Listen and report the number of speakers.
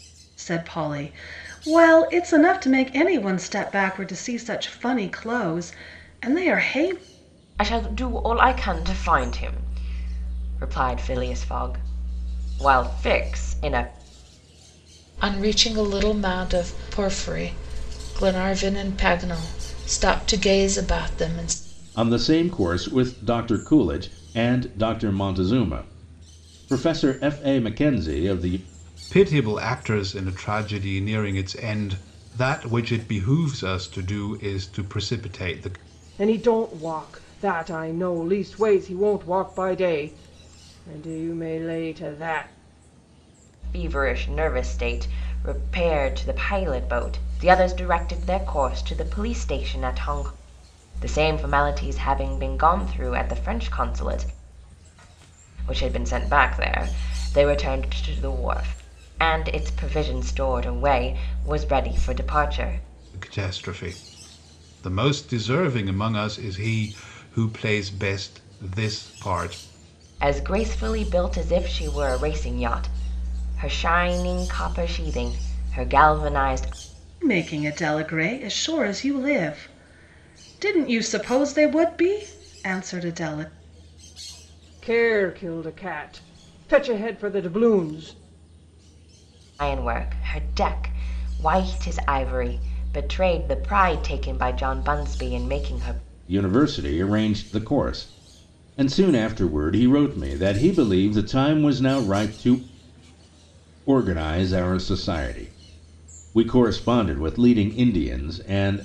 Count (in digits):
6